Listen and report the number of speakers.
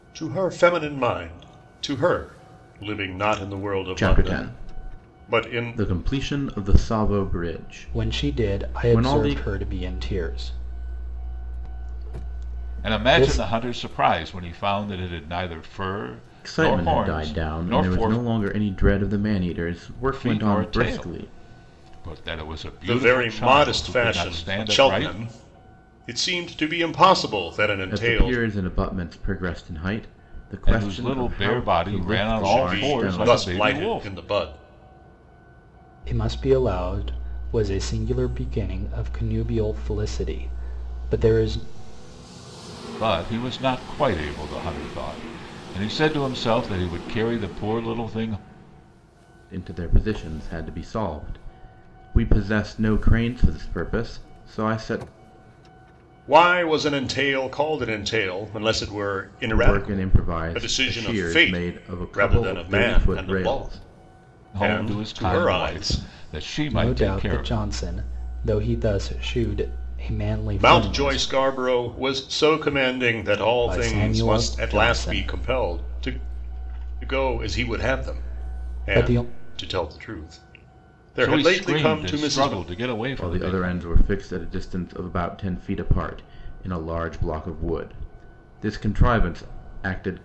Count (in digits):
4